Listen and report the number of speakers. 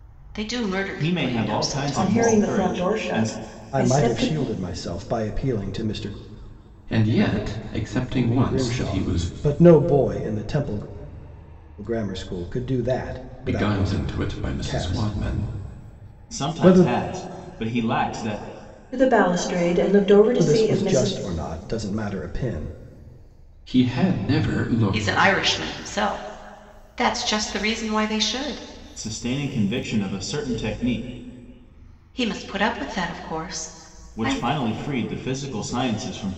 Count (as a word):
five